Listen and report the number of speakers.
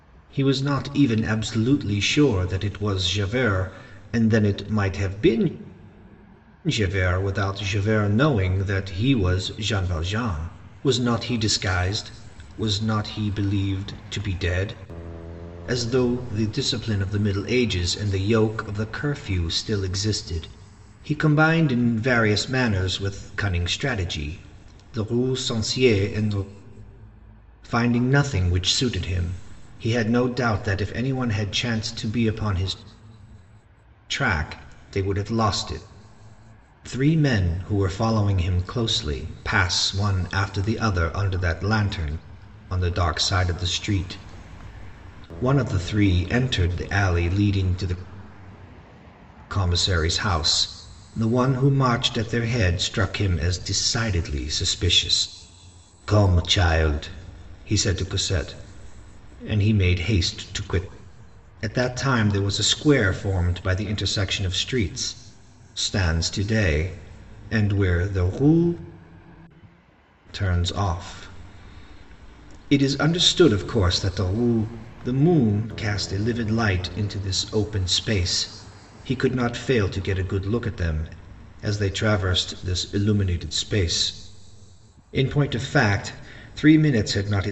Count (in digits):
1